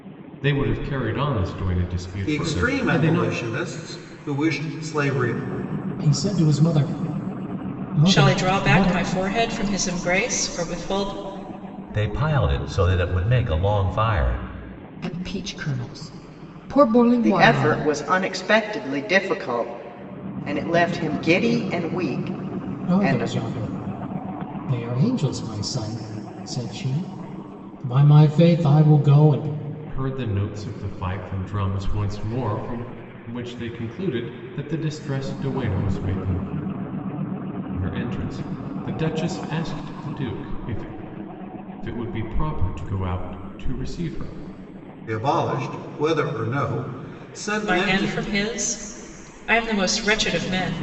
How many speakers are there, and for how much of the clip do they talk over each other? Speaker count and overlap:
seven, about 8%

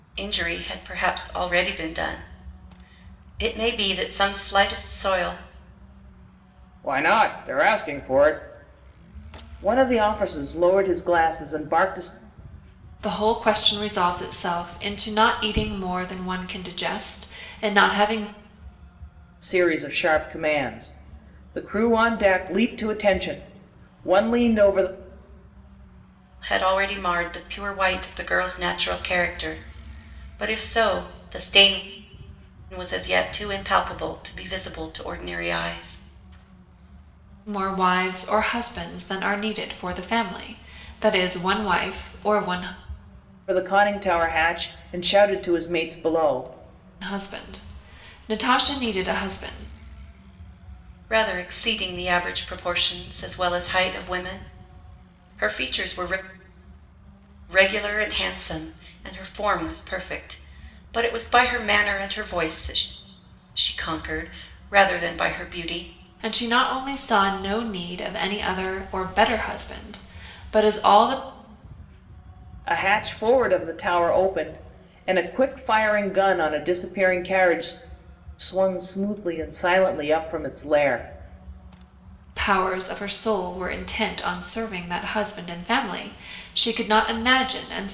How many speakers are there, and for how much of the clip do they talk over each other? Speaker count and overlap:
three, no overlap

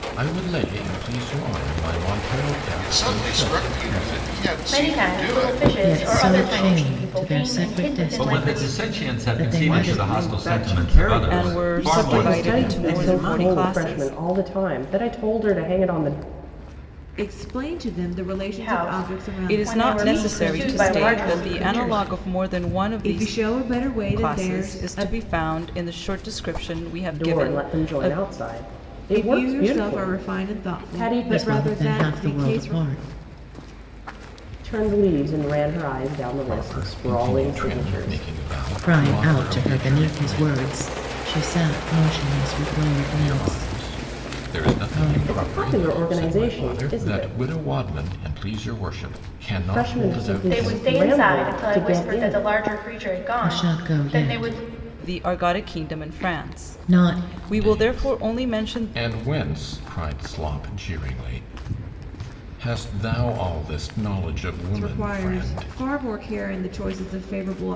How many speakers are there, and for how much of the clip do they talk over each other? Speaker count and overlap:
nine, about 57%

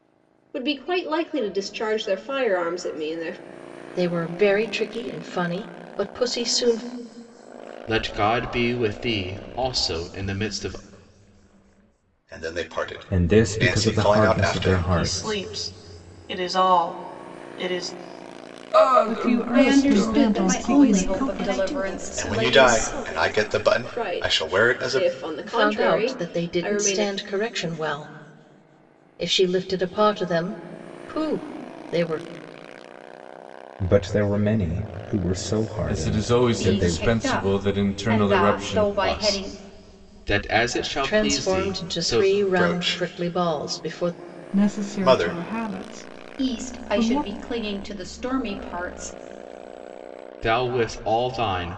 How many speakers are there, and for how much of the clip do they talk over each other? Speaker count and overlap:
ten, about 35%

